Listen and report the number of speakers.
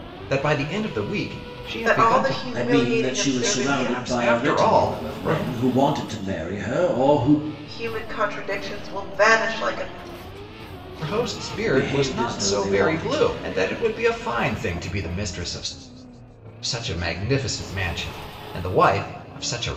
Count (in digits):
3